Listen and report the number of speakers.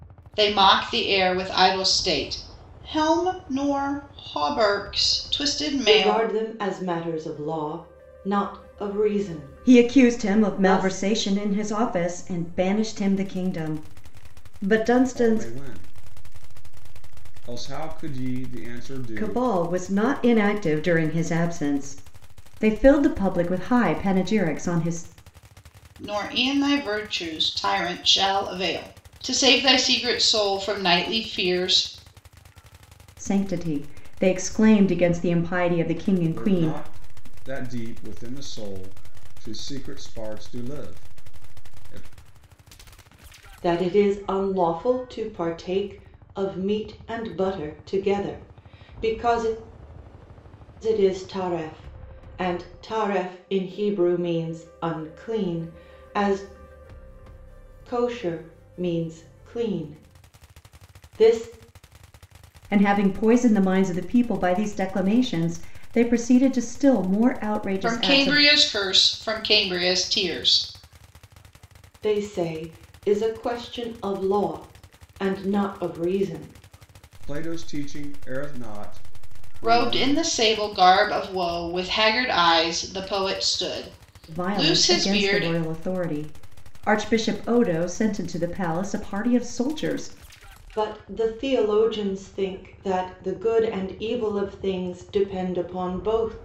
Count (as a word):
four